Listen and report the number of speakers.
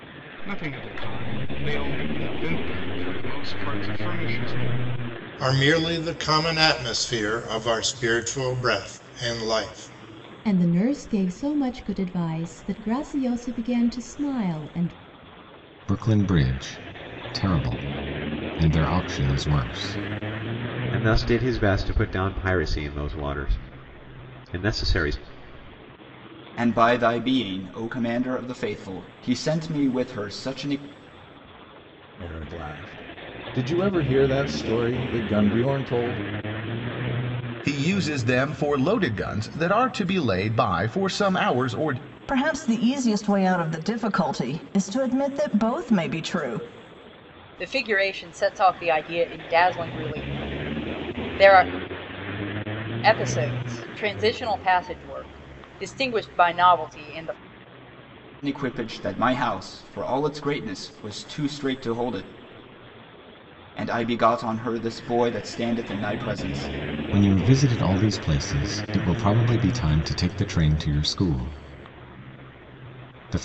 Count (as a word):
ten